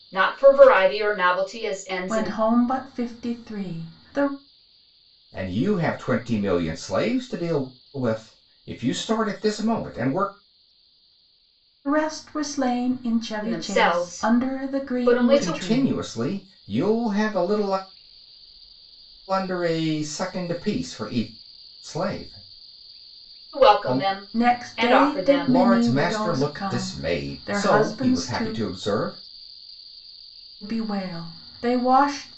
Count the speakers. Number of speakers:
three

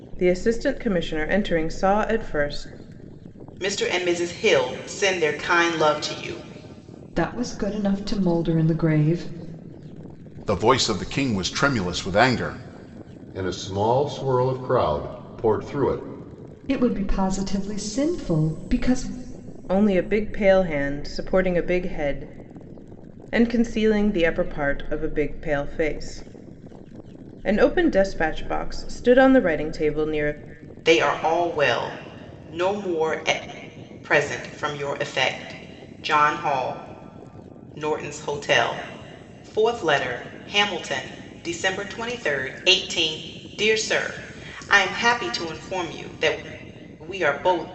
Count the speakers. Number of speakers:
five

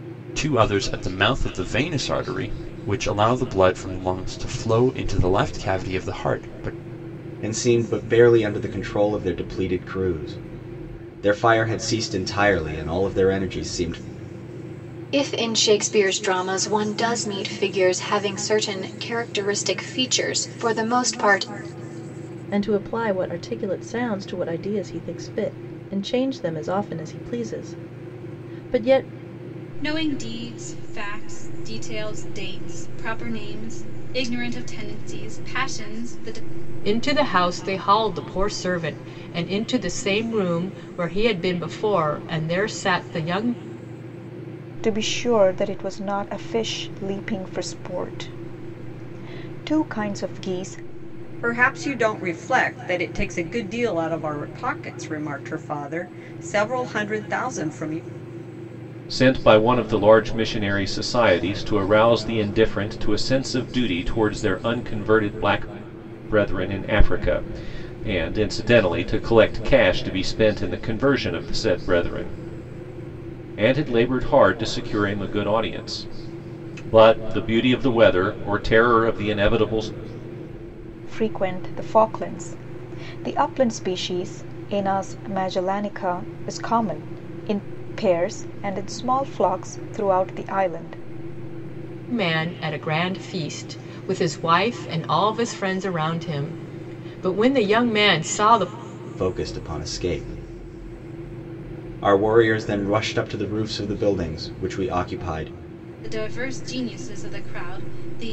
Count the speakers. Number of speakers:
nine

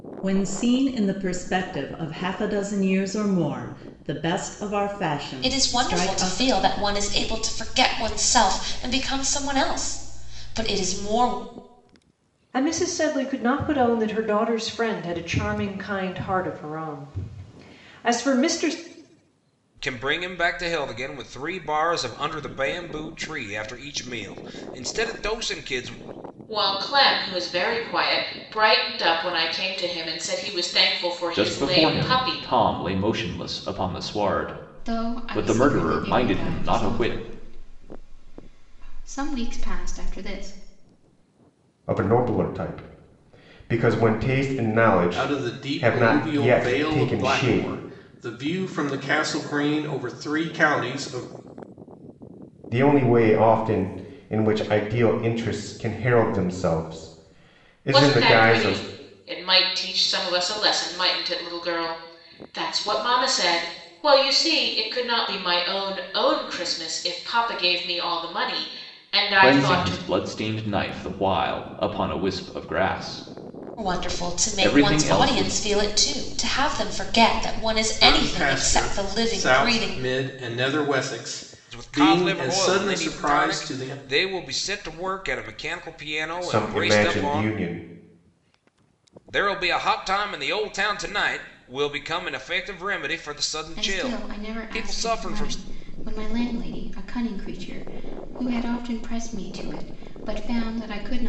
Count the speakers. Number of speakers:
nine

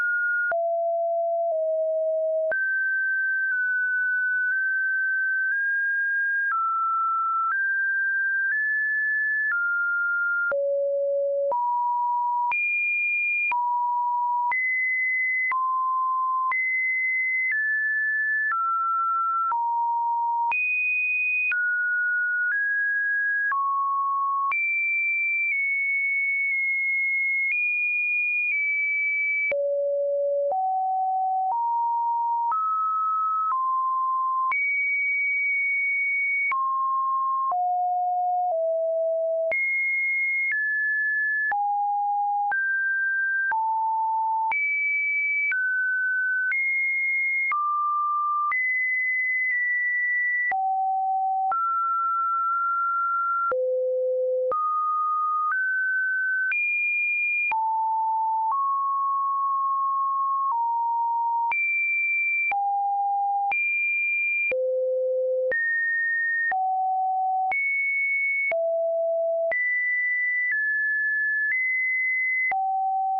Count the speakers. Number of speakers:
zero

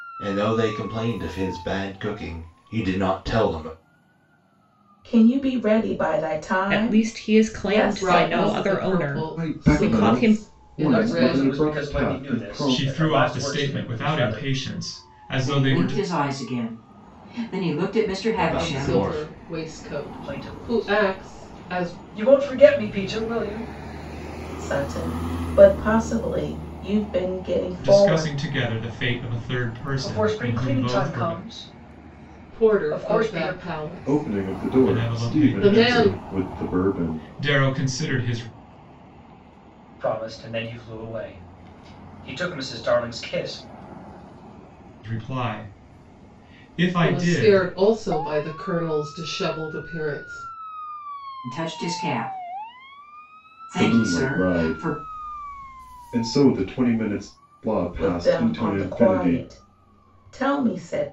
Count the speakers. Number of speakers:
eight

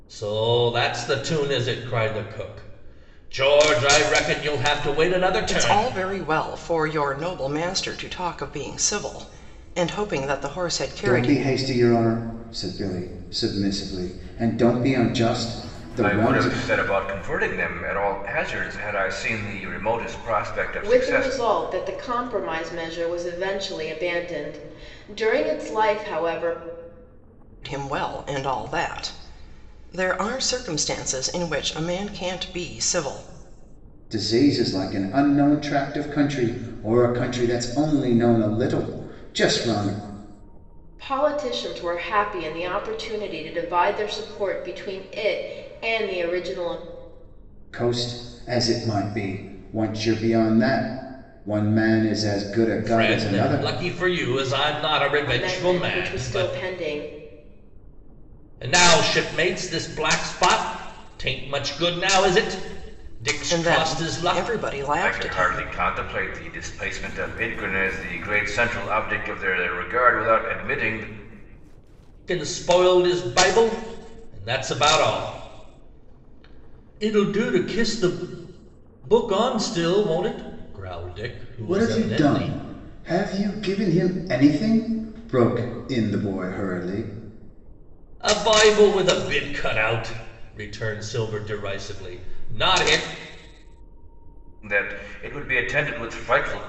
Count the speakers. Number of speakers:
five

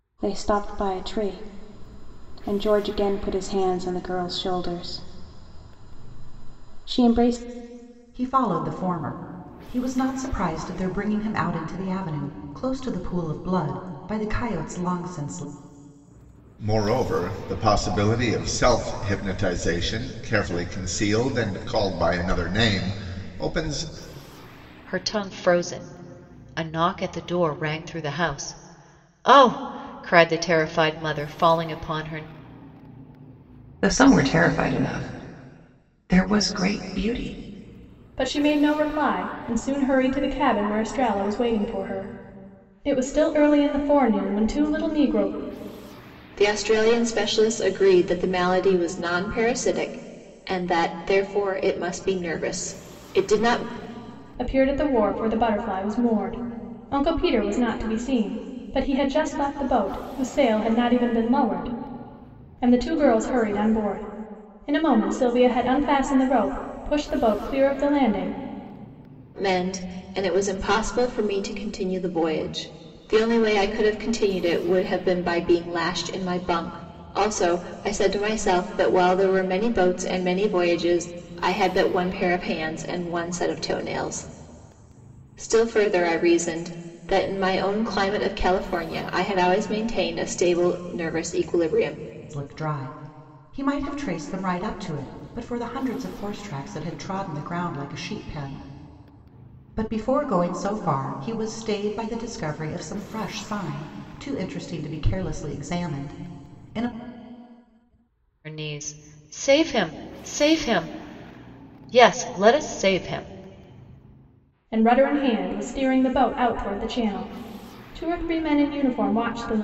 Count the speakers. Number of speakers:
seven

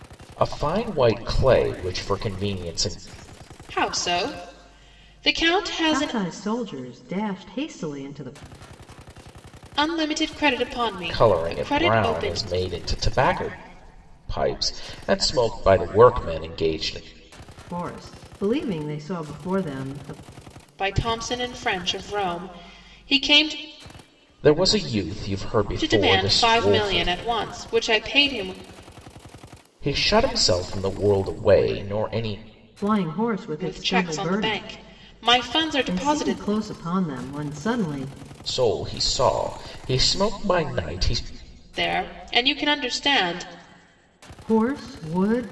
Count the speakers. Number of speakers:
three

